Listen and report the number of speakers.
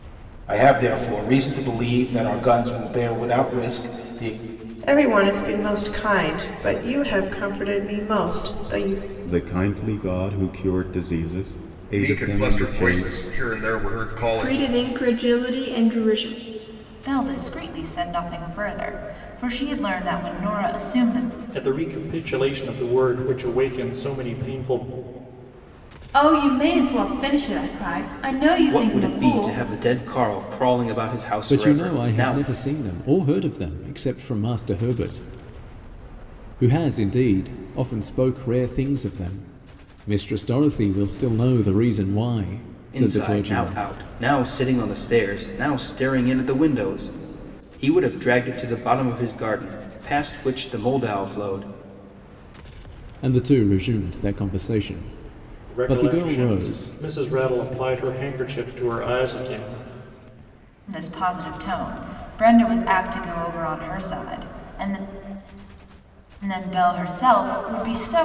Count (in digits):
10